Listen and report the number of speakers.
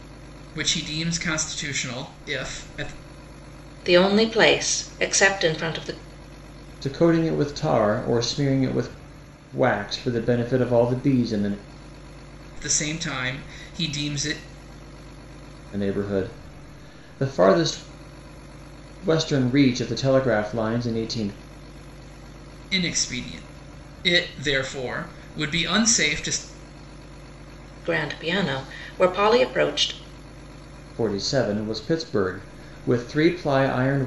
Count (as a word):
three